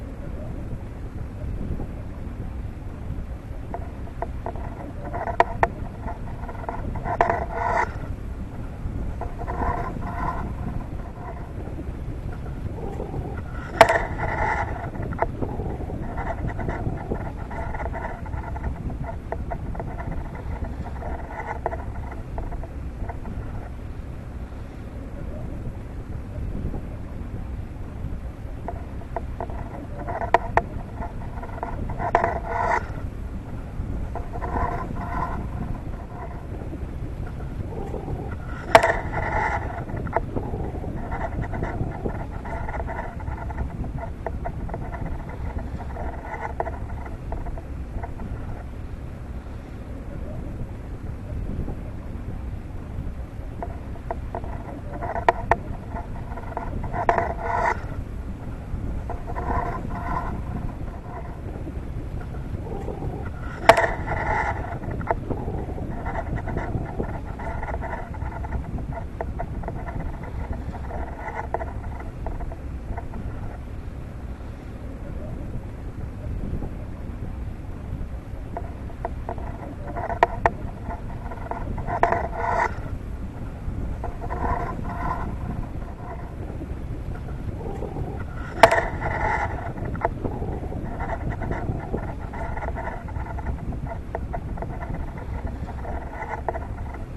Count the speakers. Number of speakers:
0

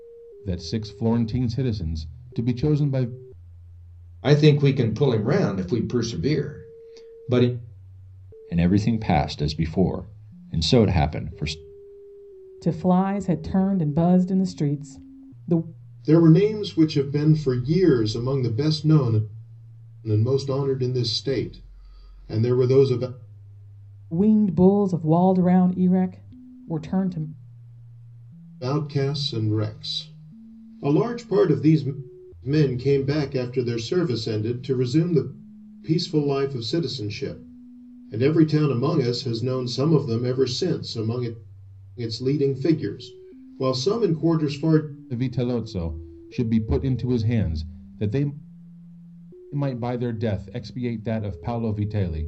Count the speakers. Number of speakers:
5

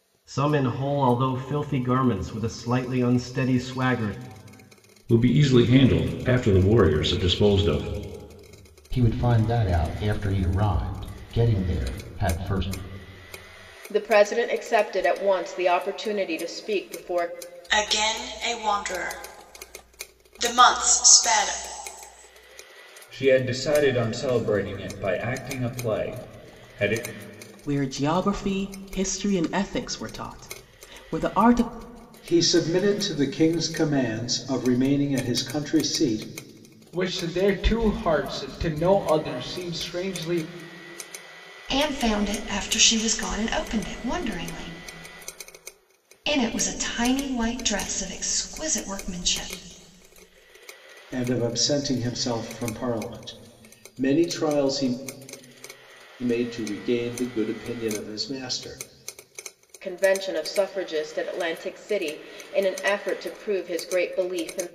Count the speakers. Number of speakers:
10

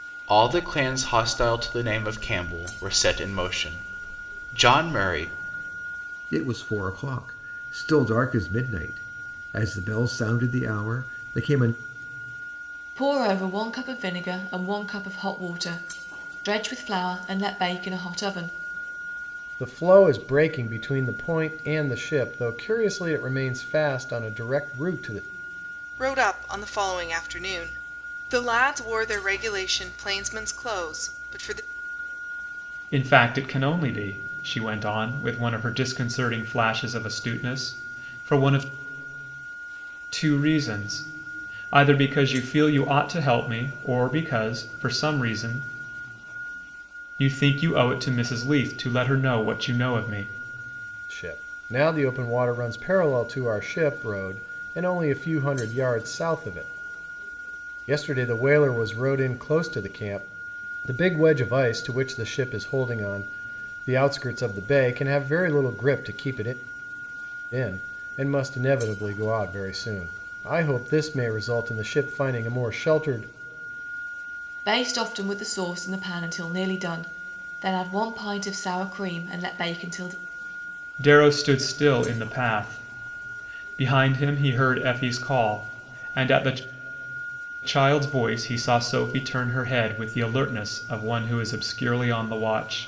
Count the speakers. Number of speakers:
6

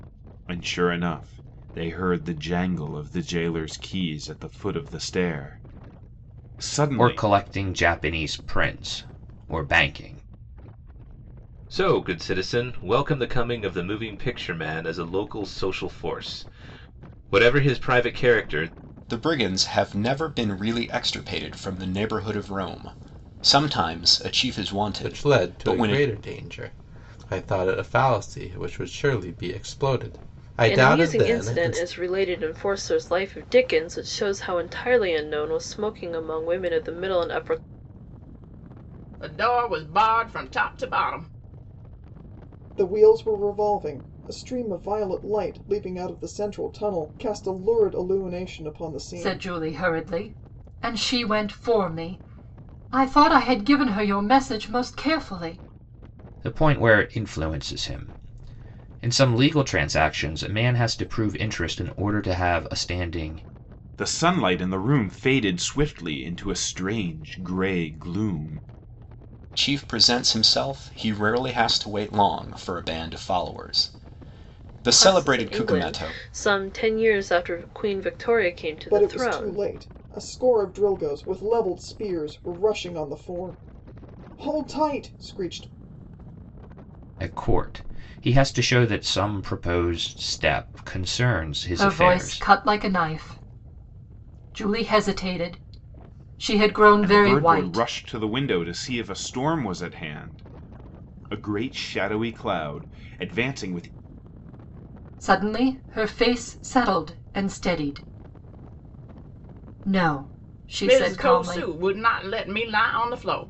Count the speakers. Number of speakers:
9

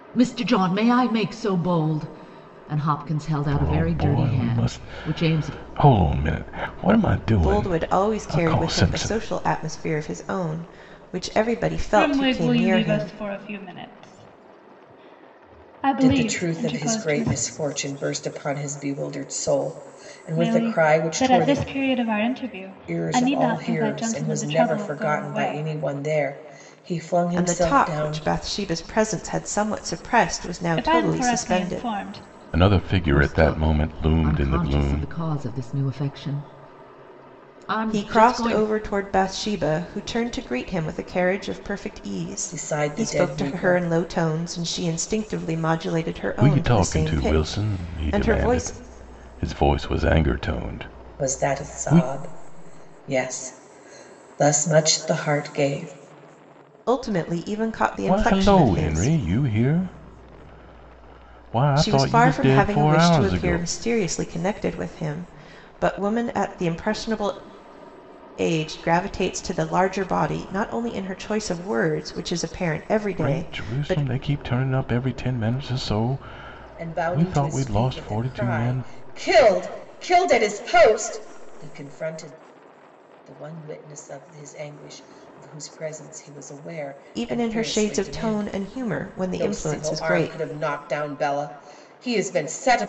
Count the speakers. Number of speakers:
5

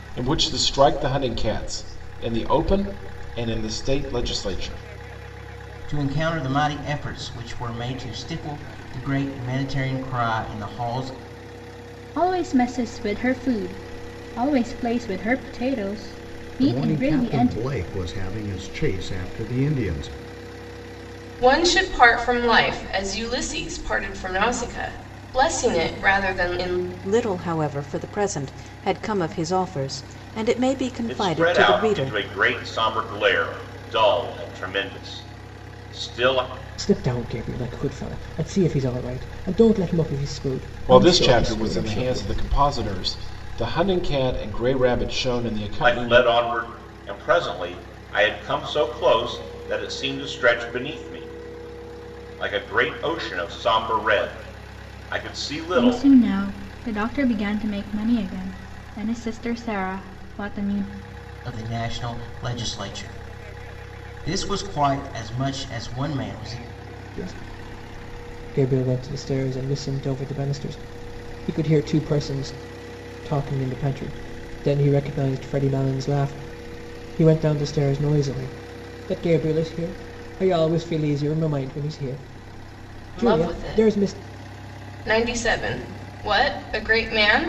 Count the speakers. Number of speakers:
8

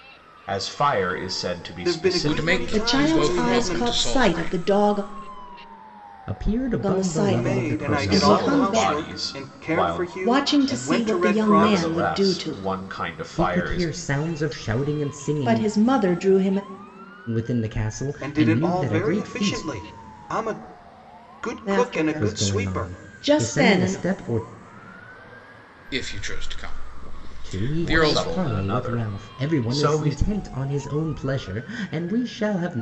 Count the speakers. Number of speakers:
5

